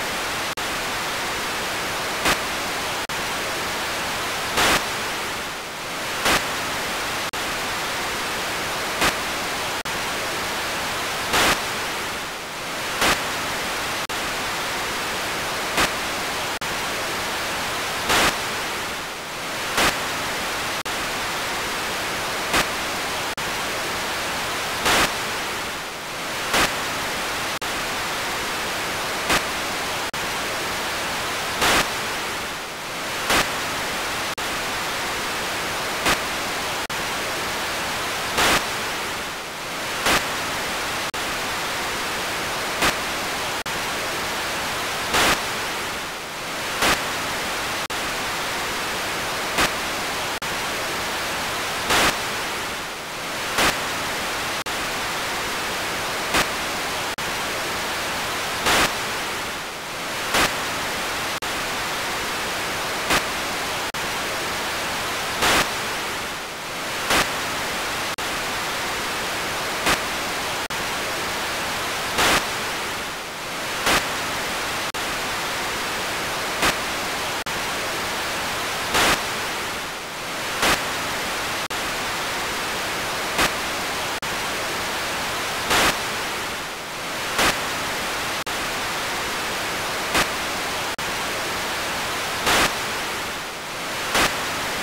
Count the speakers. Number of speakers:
0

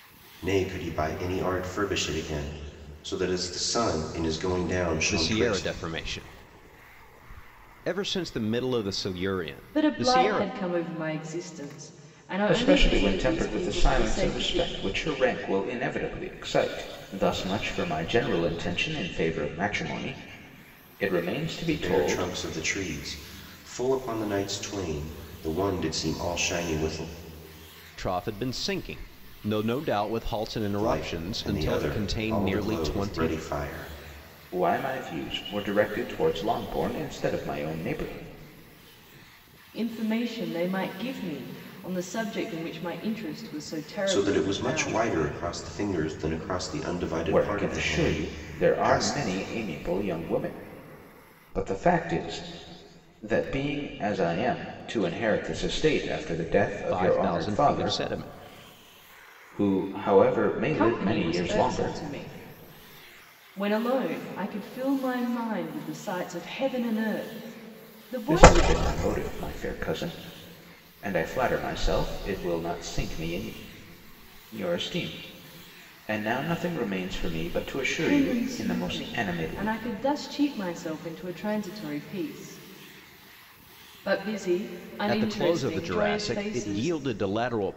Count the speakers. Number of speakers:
4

